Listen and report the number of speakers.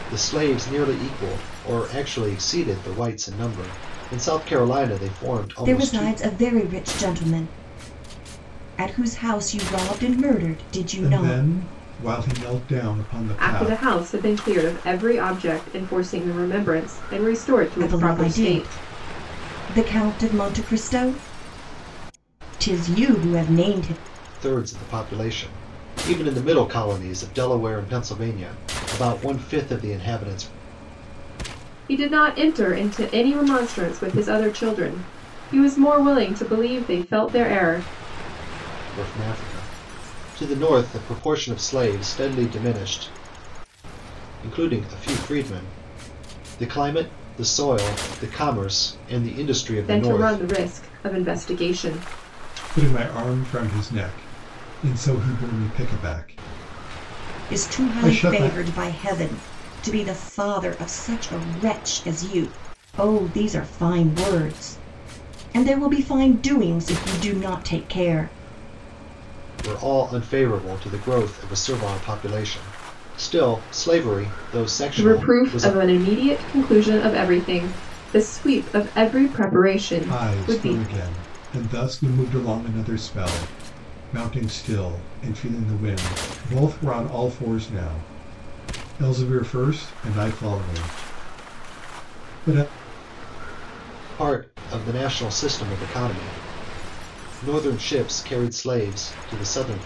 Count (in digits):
4